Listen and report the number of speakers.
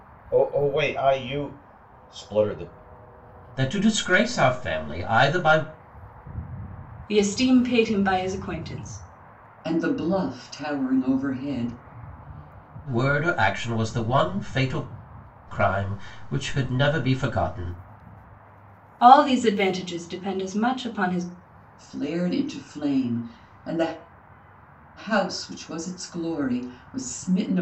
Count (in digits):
4